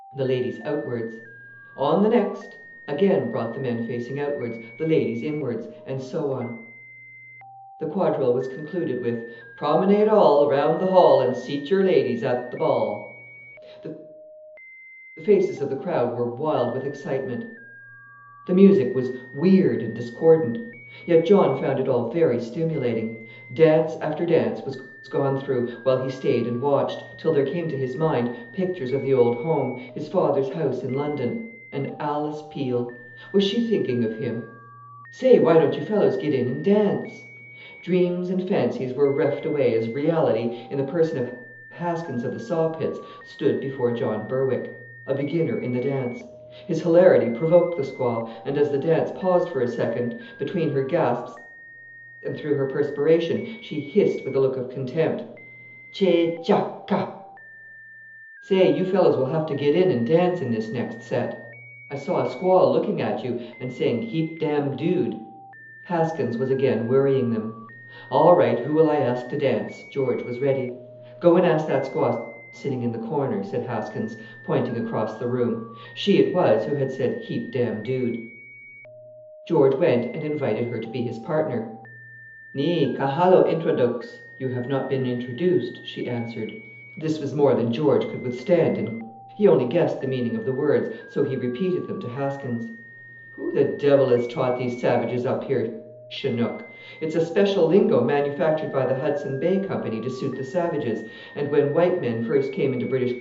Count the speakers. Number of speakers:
1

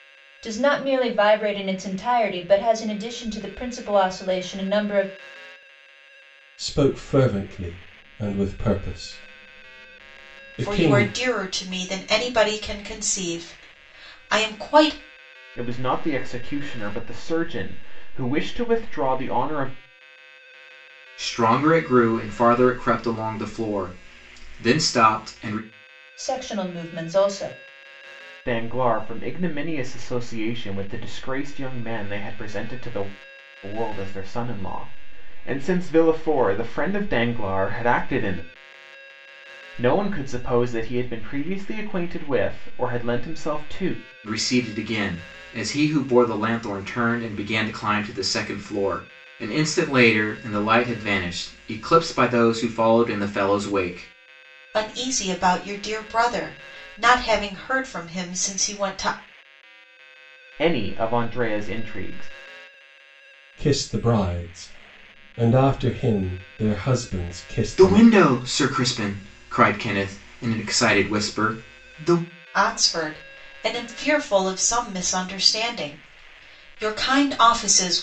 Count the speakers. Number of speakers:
5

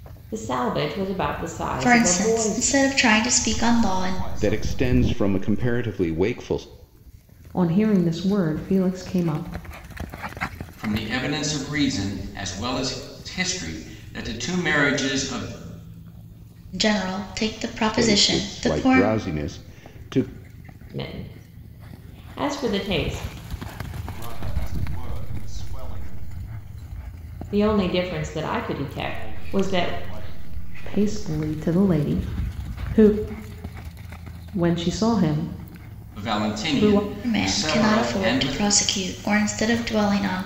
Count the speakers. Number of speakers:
6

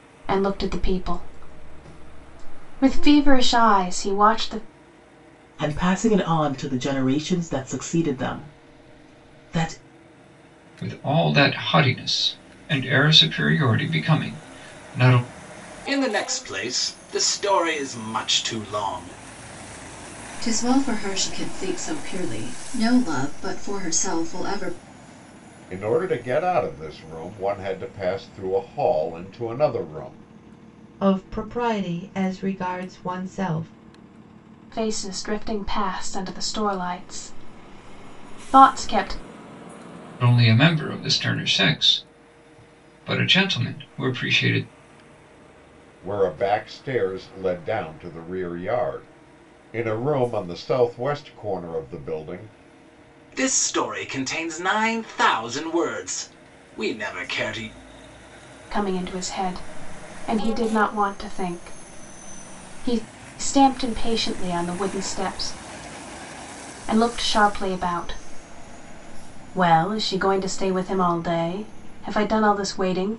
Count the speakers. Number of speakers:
7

